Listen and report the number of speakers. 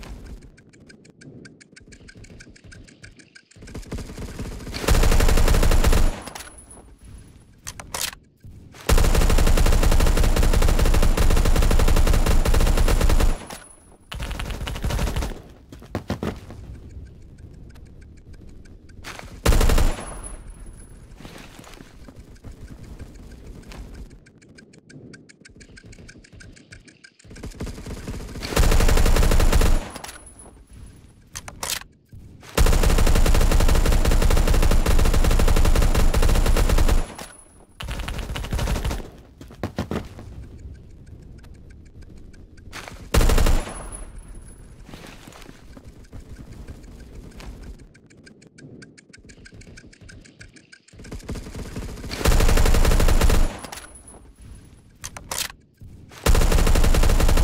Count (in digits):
0